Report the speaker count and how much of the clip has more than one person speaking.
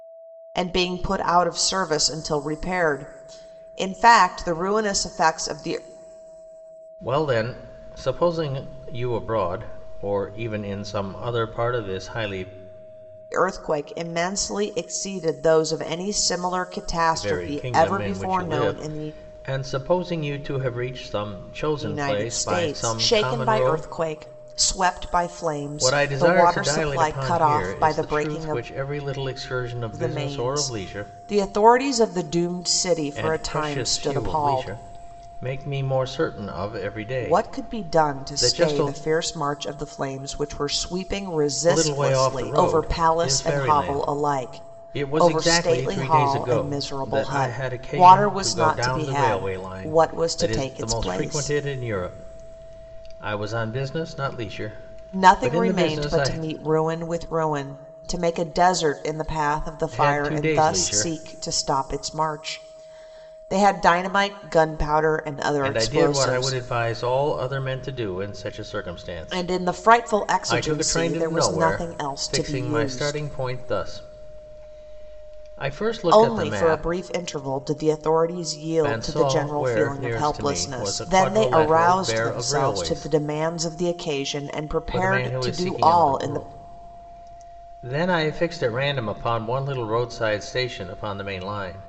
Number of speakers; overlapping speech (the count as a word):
two, about 38%